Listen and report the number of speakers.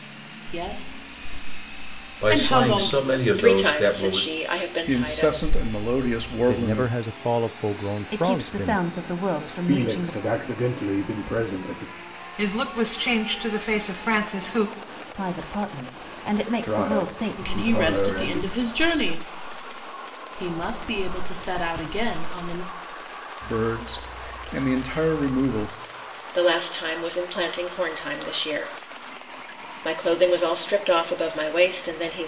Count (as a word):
eight